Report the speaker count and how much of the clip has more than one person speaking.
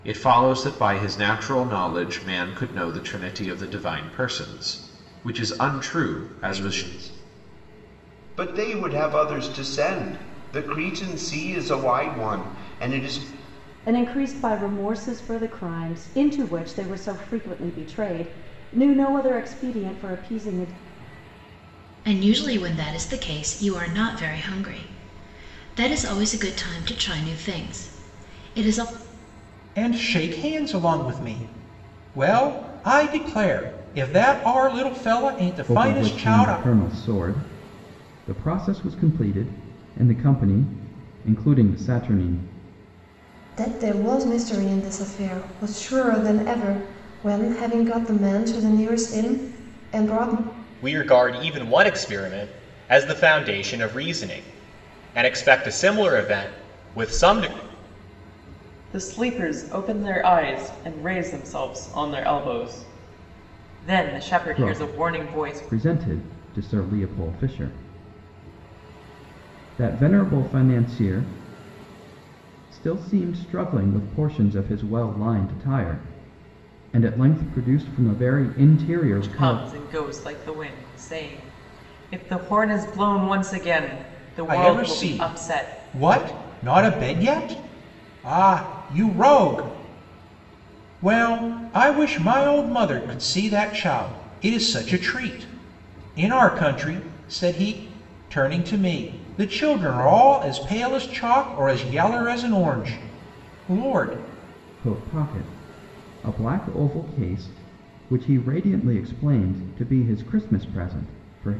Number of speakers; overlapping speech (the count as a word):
nine, about 4%